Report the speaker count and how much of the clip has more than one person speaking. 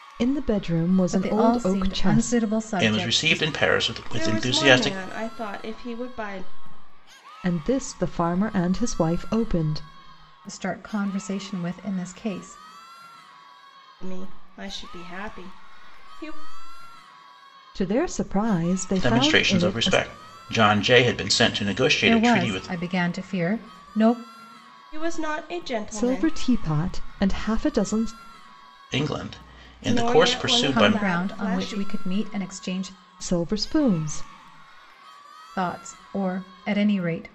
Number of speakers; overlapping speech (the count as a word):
four, about 20%